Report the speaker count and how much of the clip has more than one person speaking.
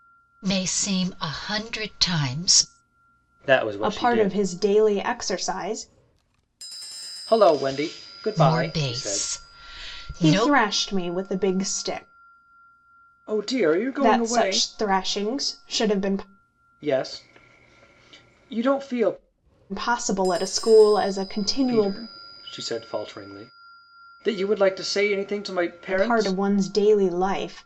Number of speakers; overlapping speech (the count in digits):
3, about 12%